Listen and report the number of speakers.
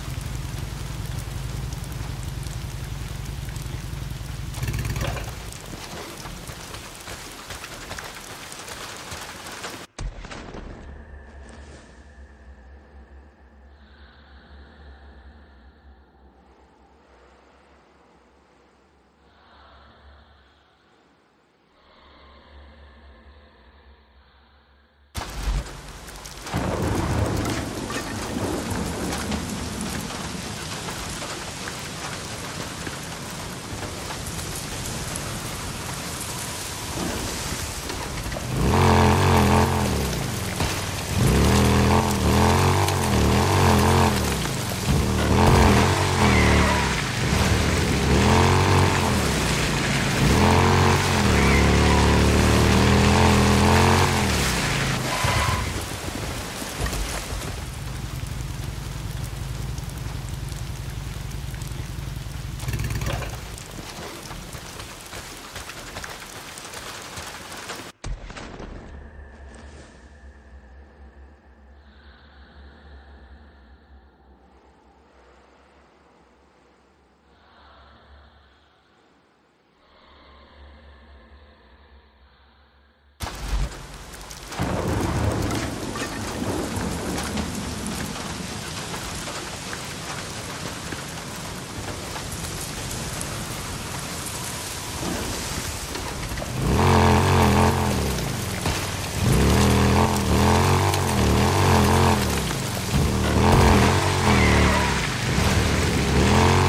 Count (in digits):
0